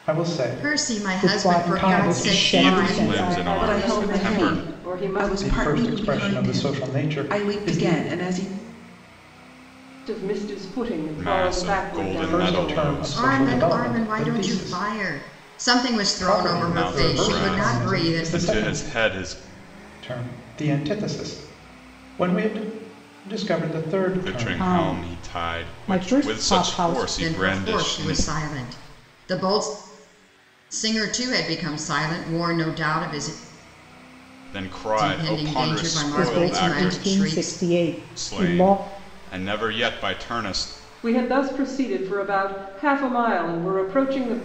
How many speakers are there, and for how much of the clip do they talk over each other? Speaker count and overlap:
6, about 48%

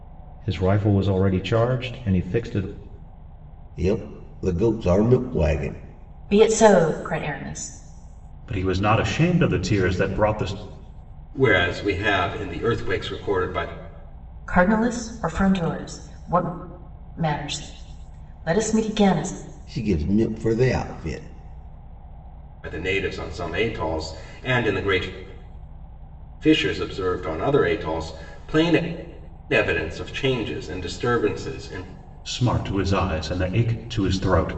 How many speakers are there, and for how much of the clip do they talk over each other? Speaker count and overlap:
5, no overlap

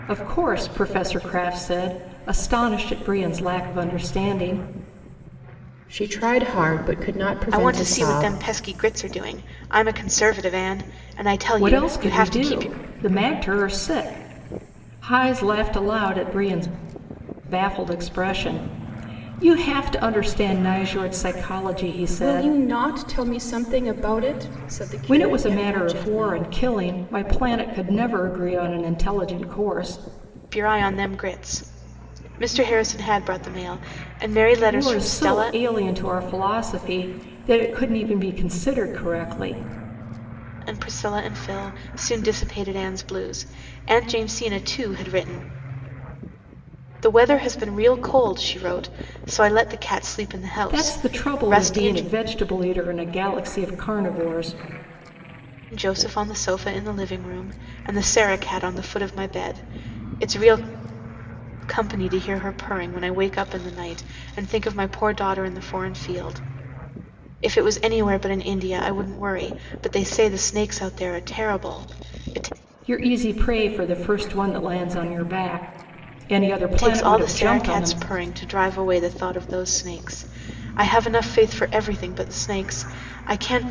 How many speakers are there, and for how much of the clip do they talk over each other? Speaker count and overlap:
3, about 9%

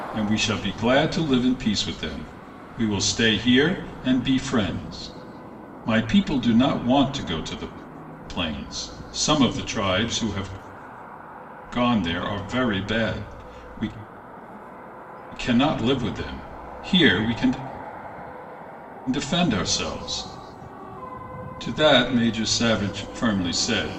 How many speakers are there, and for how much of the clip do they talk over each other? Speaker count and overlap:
1, no overlap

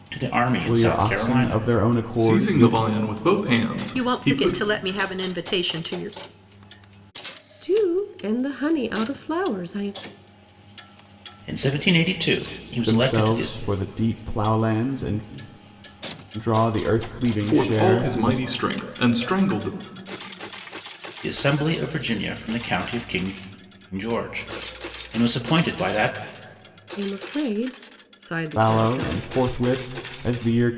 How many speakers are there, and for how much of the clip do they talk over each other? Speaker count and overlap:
5, about 17%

